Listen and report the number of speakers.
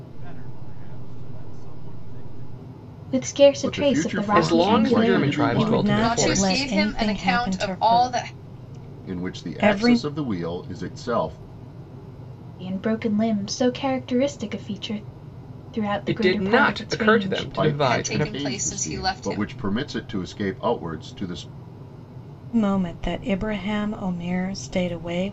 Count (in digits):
6